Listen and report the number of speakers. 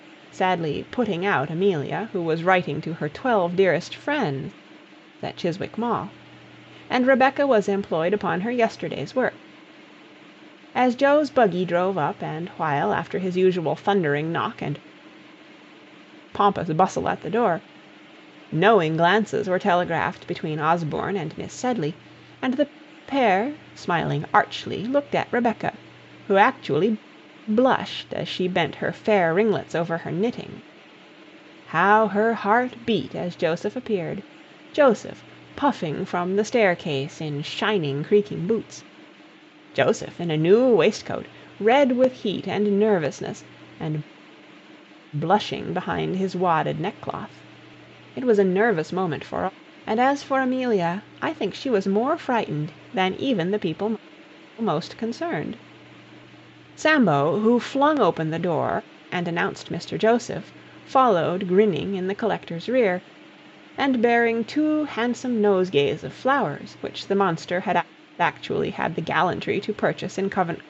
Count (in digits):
1